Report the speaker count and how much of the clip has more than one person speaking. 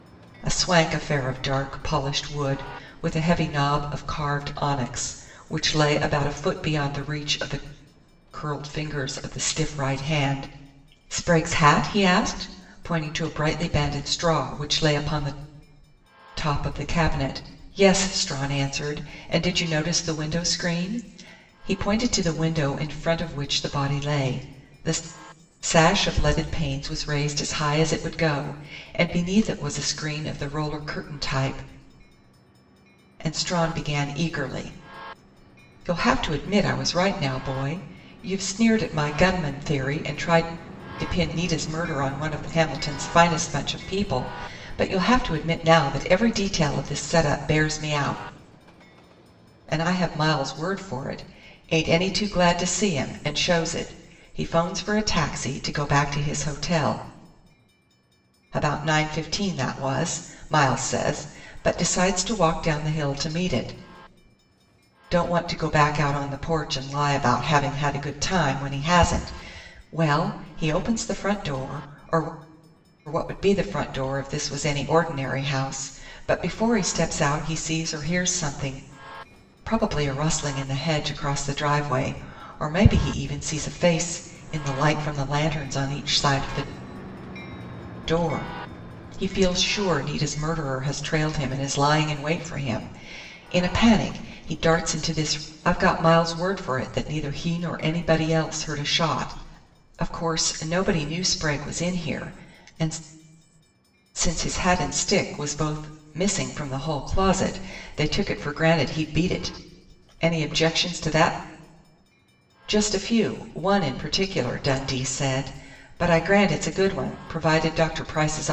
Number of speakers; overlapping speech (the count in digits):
1, no overlap